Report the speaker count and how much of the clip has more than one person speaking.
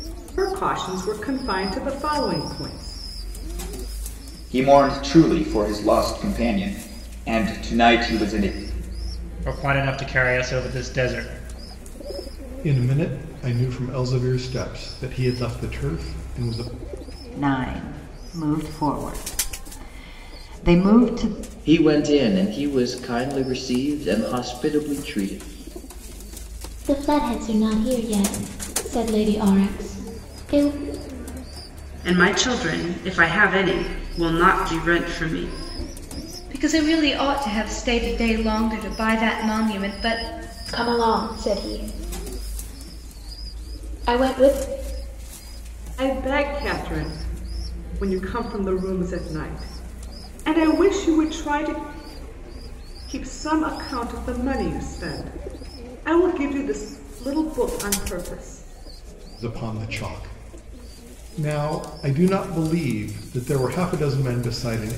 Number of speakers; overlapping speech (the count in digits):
10, no overlap